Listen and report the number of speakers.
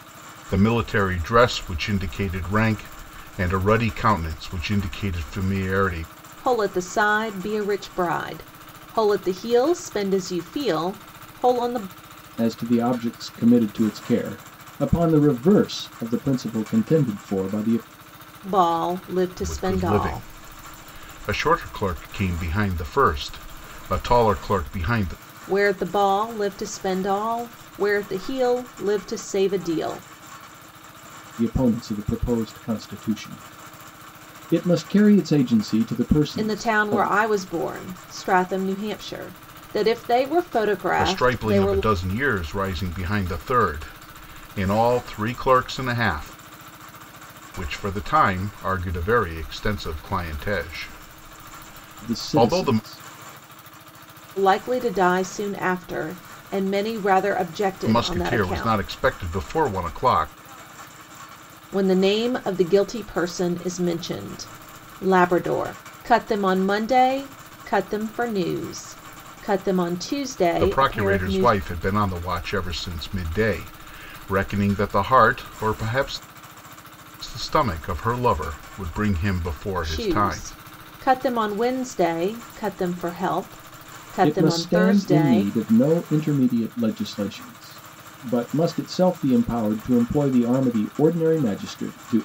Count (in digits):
3